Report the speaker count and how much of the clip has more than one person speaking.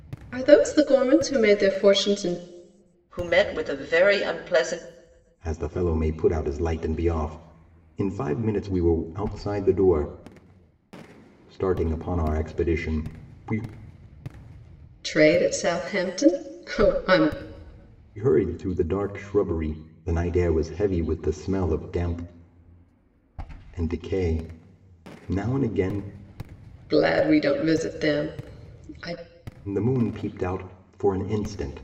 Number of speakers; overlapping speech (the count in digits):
3, no overlap